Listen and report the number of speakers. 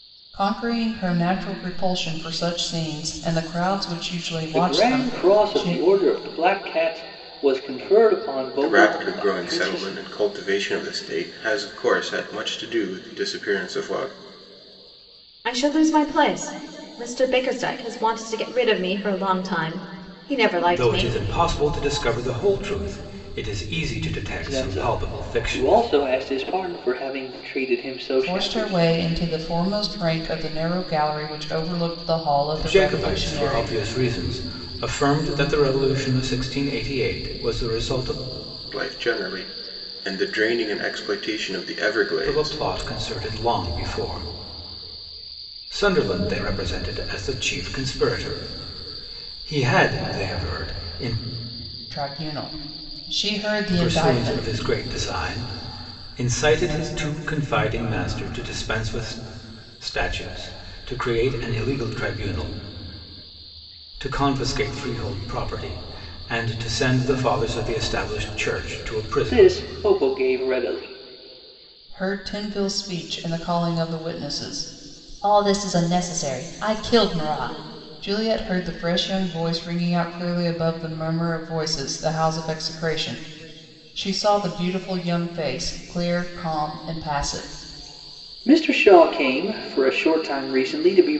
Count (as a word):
five